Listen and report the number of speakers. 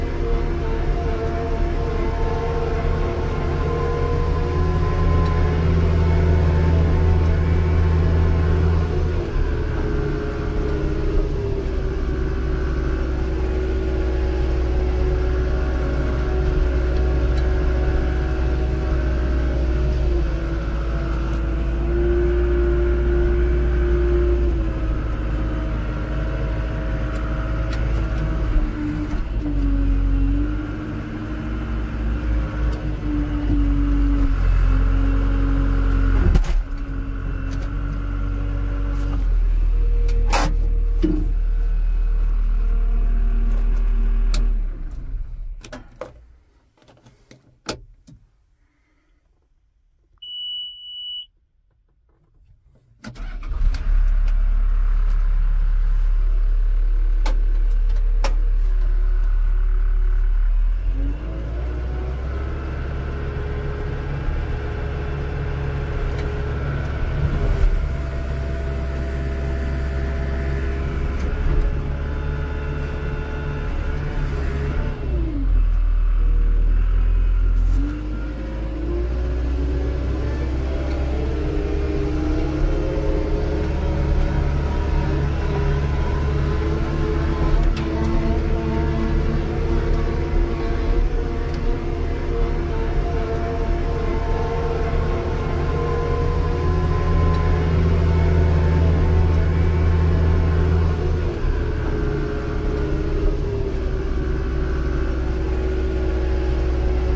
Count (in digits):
0